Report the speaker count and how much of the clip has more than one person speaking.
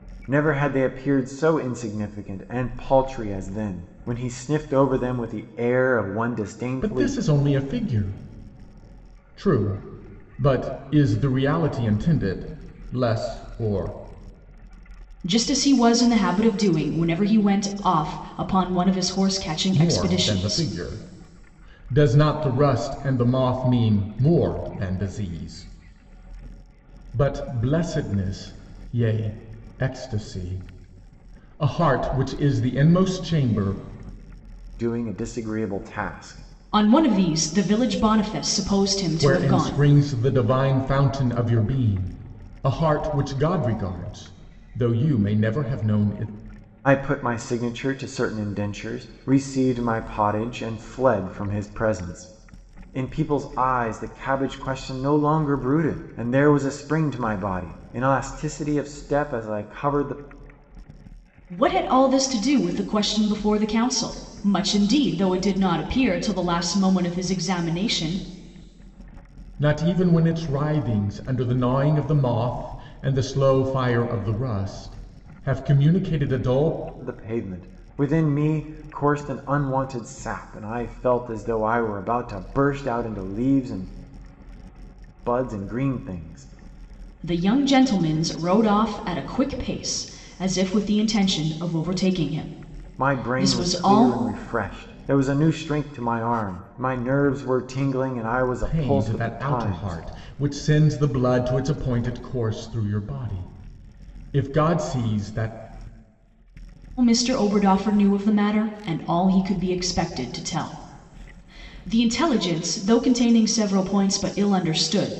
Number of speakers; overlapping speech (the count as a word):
three, about 4%